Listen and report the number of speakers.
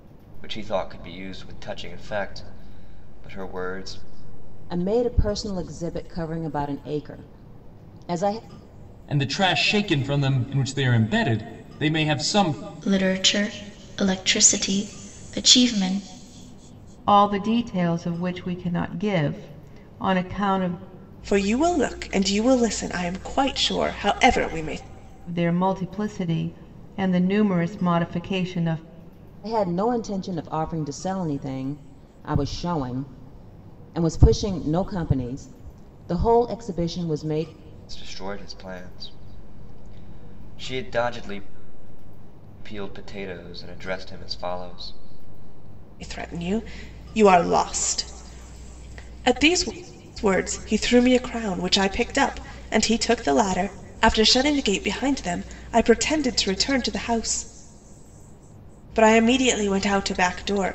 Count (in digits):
6